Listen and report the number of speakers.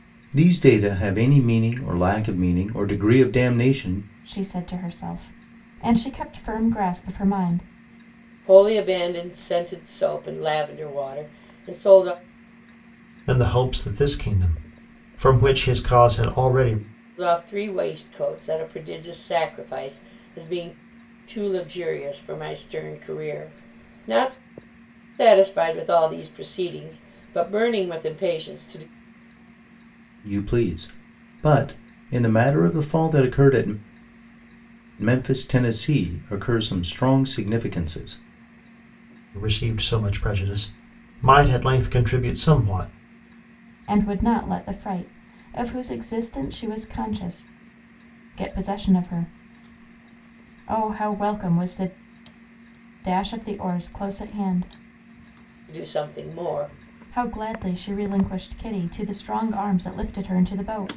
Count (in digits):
4